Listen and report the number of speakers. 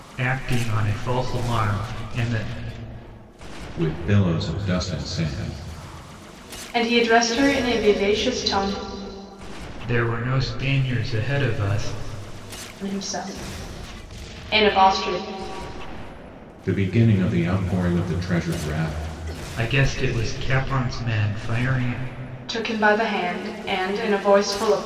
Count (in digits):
3